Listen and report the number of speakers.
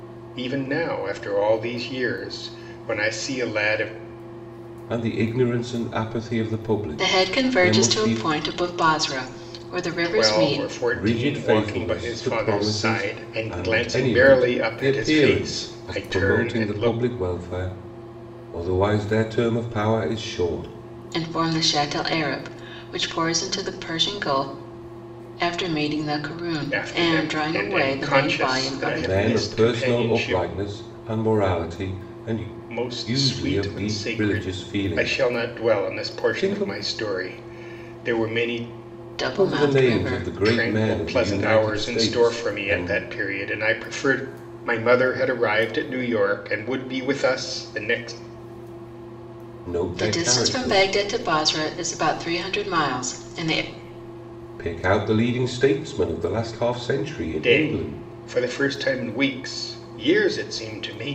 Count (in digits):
3